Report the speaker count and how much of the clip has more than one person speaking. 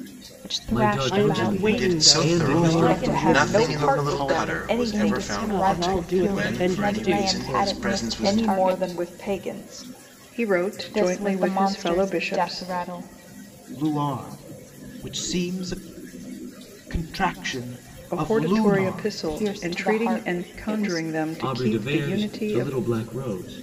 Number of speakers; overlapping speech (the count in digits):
6, about 61%